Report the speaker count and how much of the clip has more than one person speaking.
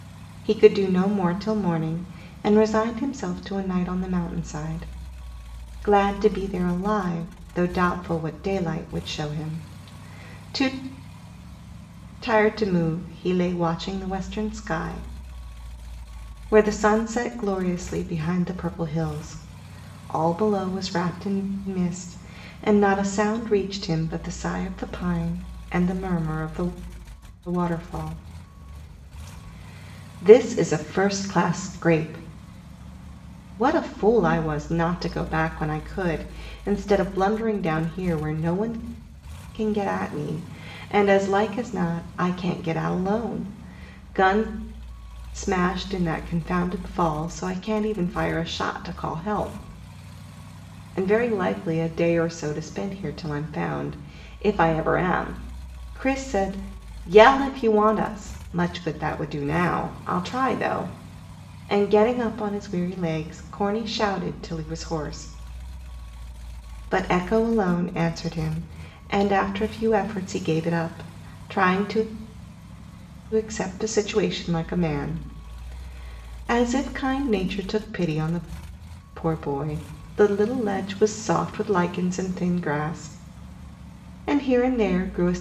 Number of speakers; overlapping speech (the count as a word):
one, no overlap